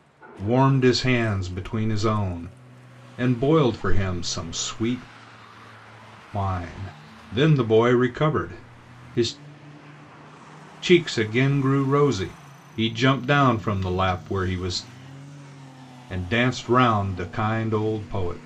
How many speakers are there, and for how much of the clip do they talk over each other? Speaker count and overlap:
1, no overlap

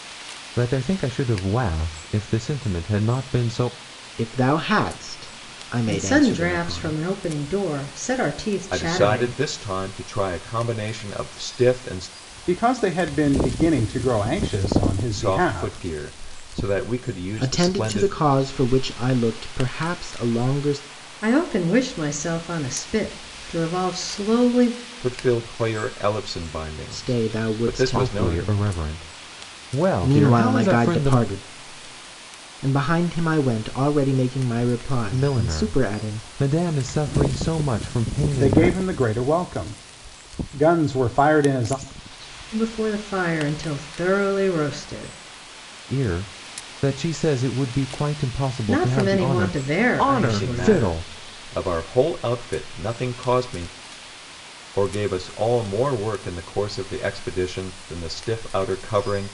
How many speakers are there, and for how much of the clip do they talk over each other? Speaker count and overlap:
5, about 17%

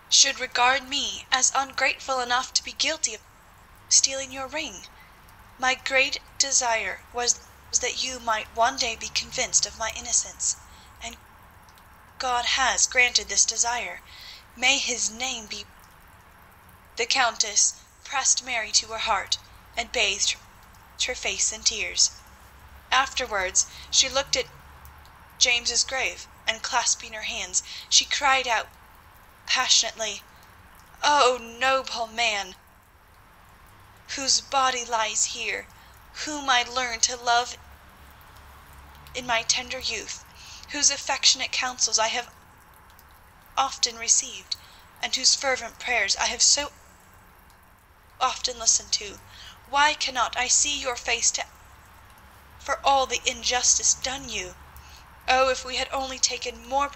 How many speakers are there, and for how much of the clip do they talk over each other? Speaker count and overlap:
1, no overlap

